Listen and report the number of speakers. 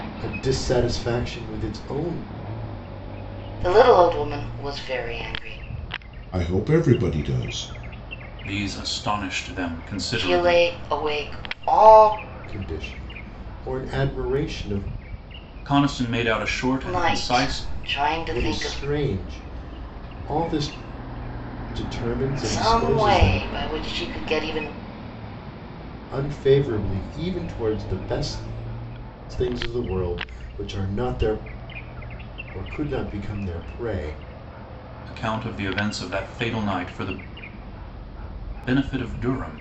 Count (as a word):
four